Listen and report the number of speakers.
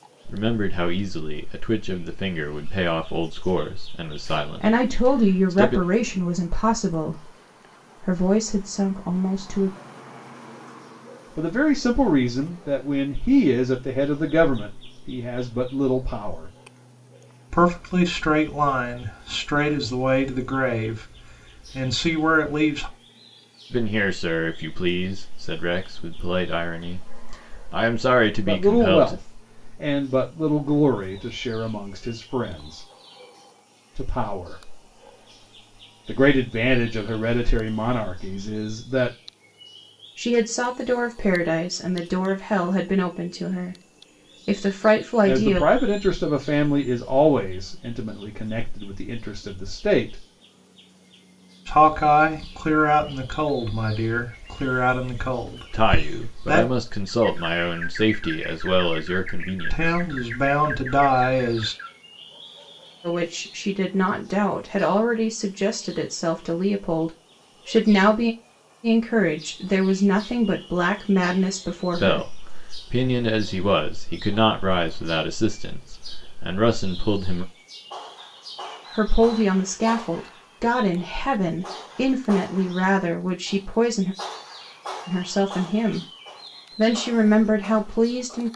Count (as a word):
four